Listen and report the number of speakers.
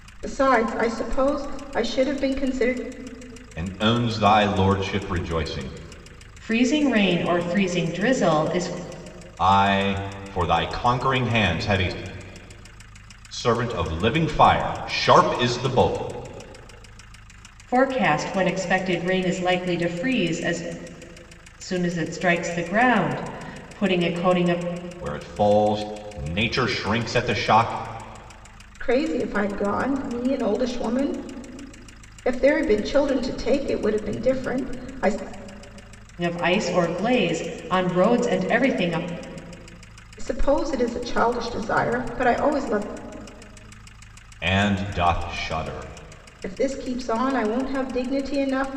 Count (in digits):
3